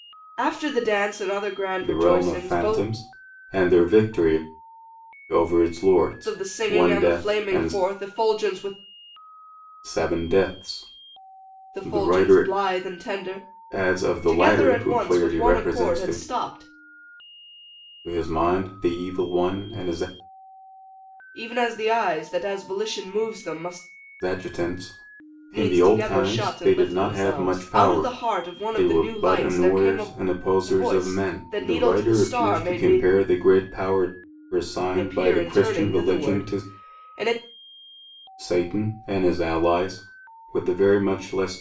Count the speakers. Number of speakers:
2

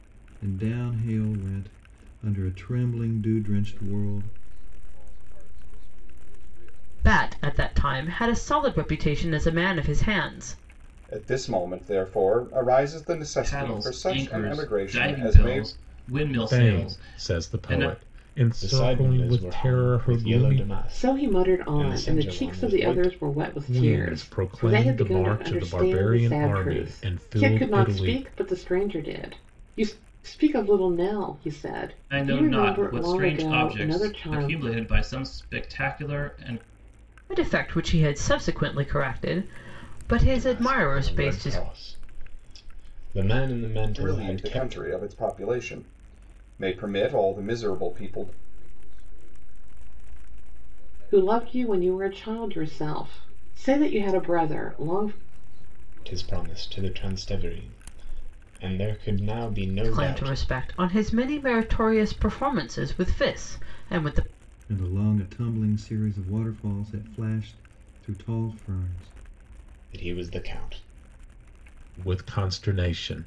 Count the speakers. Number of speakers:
8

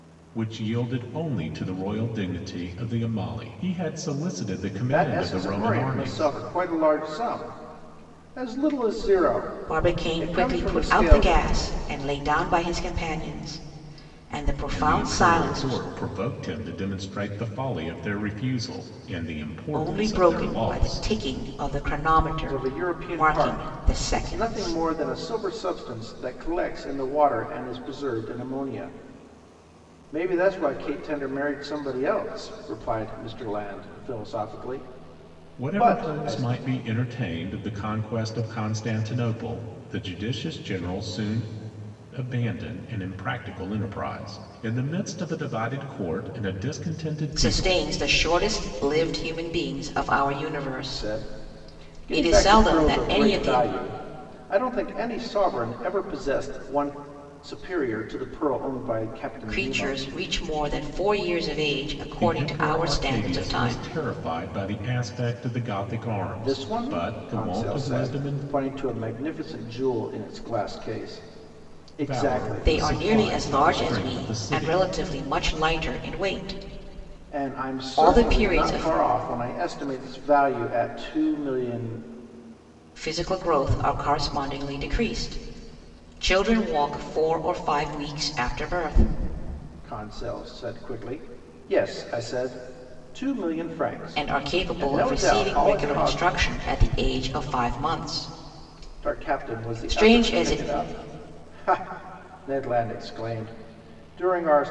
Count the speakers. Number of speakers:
3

